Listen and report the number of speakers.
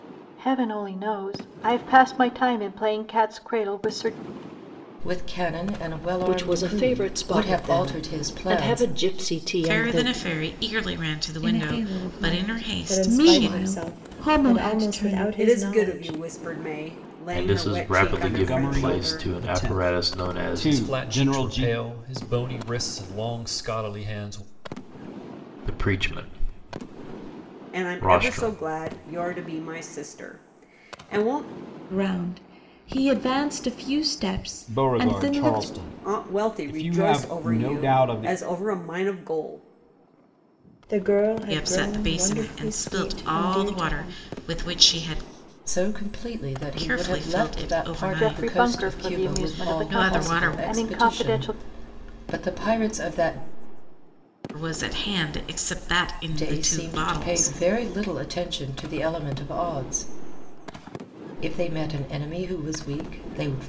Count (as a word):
ten